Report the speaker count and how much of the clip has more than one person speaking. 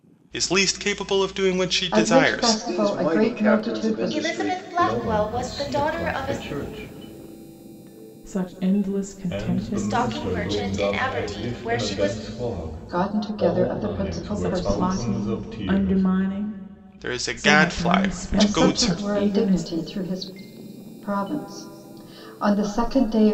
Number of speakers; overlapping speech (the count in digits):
6, about 56%